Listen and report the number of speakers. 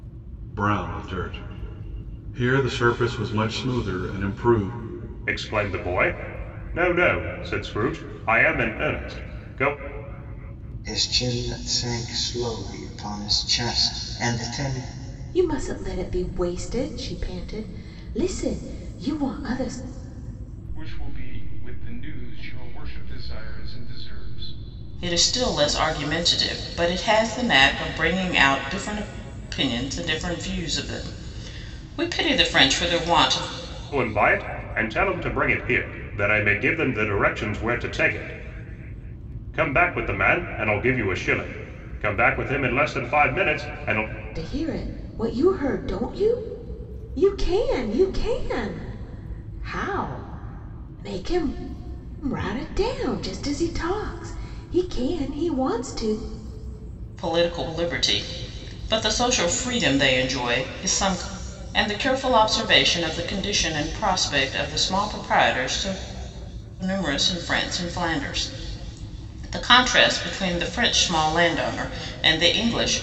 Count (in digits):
6